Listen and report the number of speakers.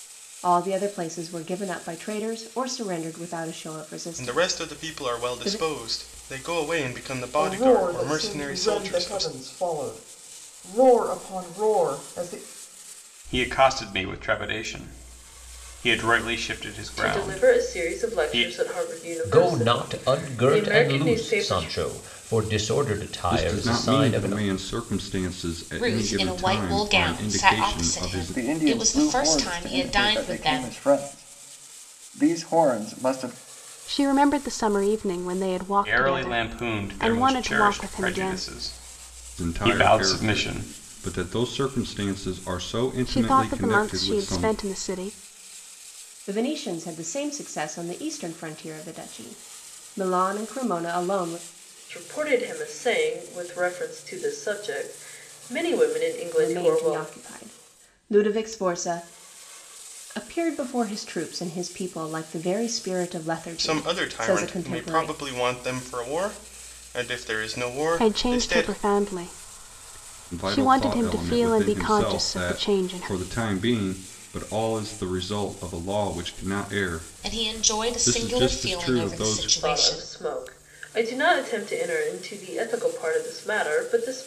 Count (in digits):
10